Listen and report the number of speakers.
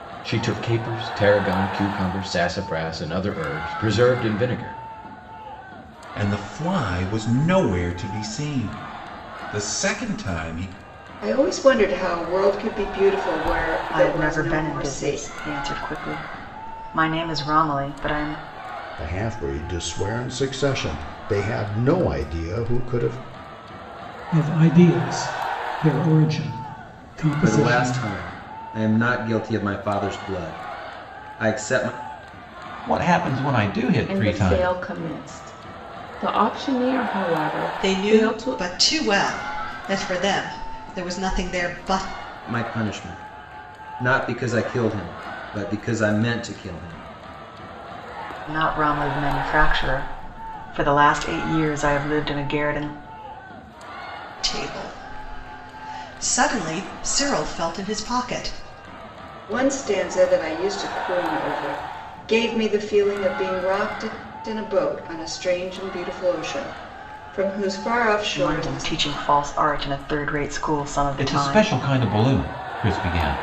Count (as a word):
ten